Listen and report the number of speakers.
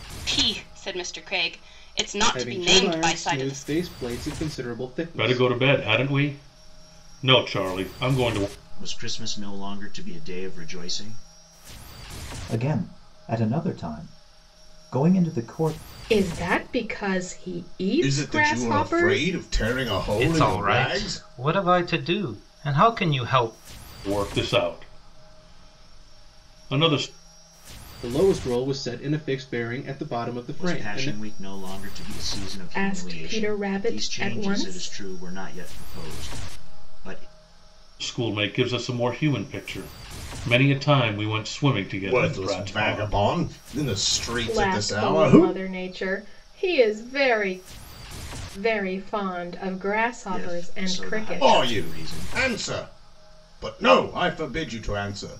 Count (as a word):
eight